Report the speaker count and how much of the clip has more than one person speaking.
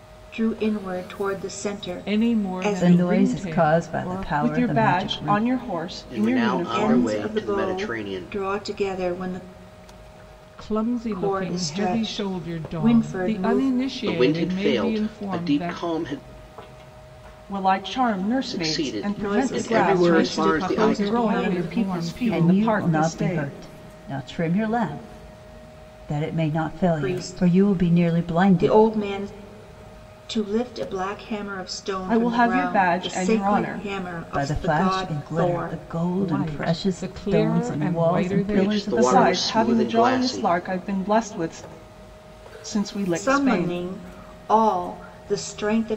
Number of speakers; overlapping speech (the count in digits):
5, about 55%